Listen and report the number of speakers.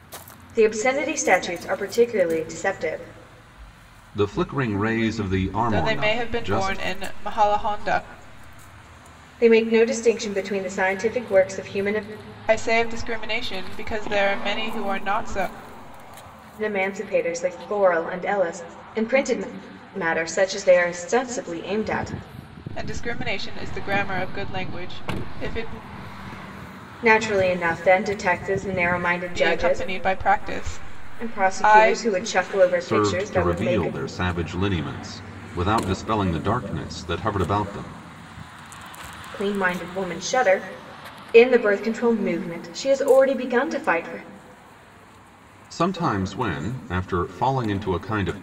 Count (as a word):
three